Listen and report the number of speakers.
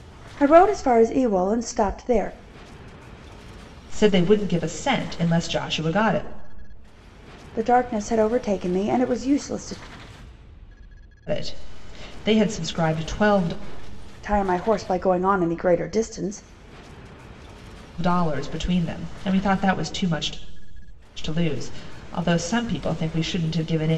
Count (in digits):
2